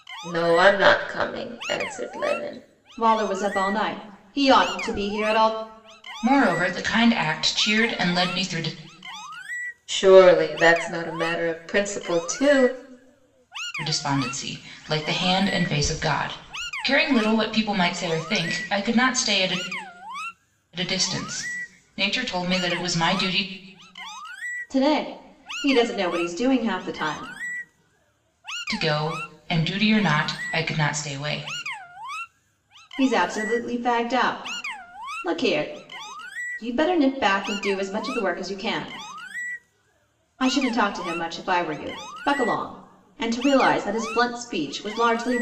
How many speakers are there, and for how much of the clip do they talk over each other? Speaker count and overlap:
3, no overlap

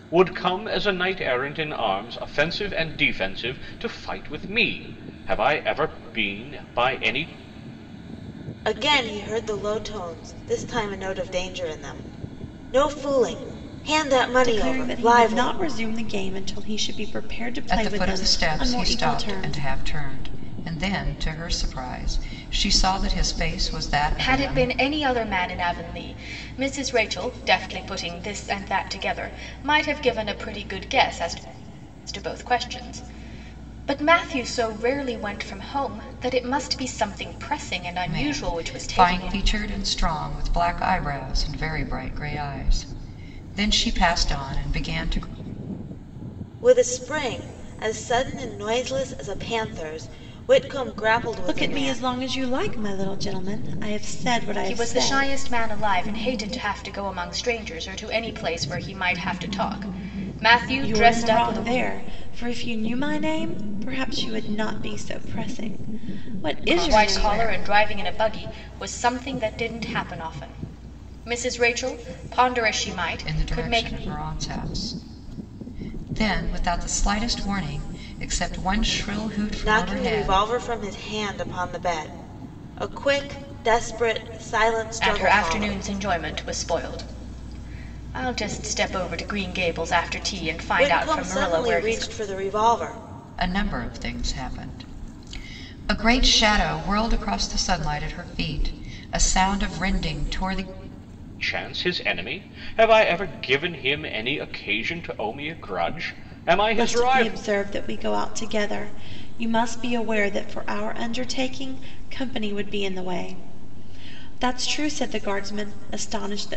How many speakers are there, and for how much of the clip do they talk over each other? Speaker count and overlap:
5, about 11%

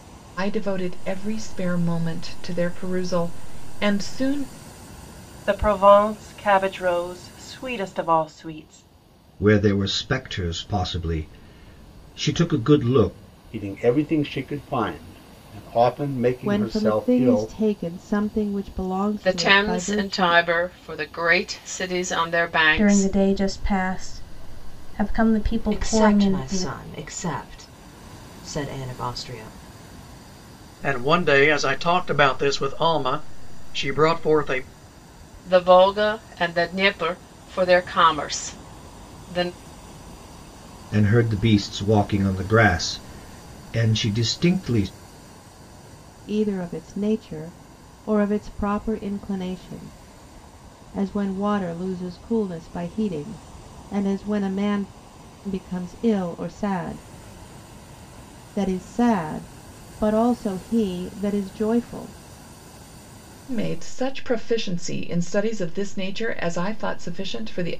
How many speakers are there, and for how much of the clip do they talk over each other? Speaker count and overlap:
9, about 6%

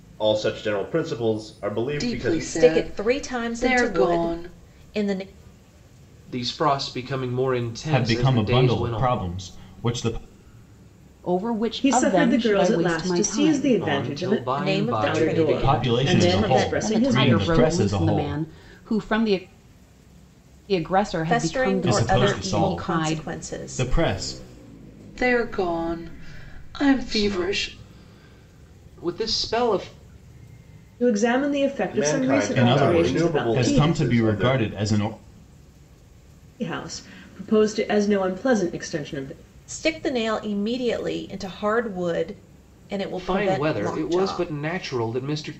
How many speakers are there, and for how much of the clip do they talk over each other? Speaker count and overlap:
7, about 38%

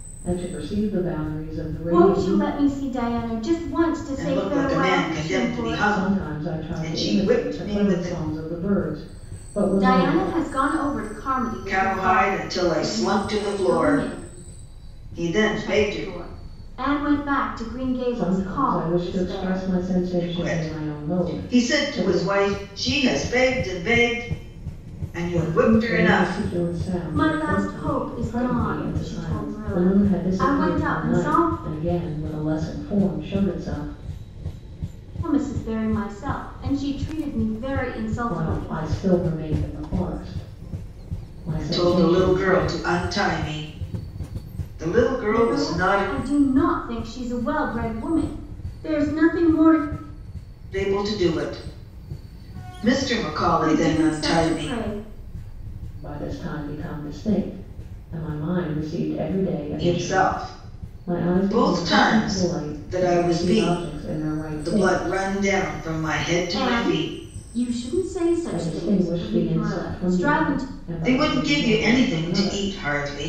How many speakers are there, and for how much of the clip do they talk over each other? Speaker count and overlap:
3, about 41%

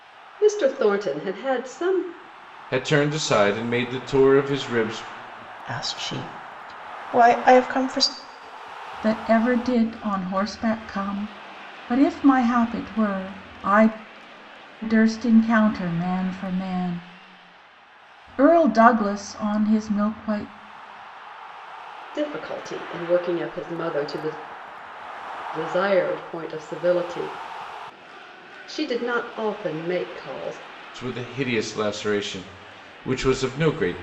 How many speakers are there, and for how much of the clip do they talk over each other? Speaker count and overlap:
4, no overlap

